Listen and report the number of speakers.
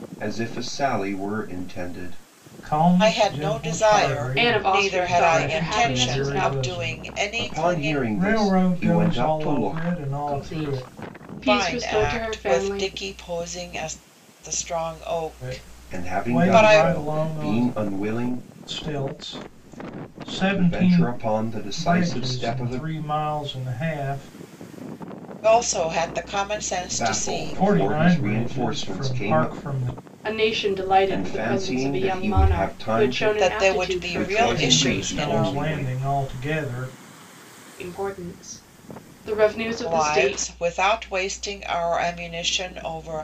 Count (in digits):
4